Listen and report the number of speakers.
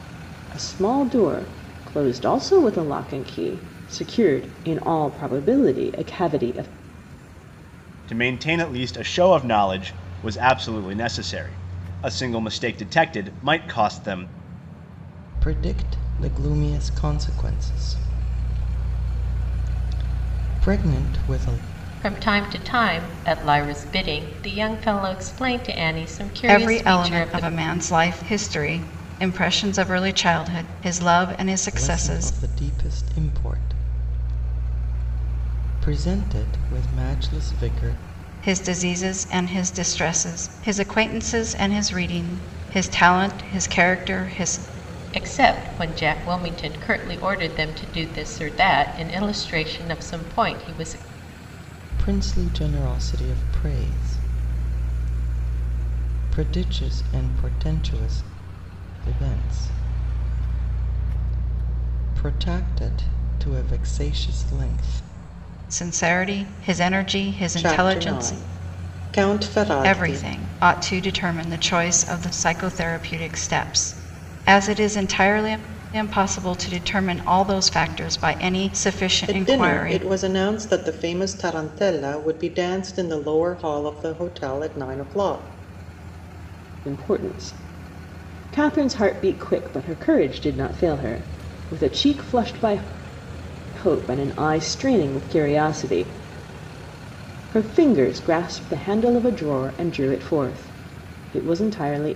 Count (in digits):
5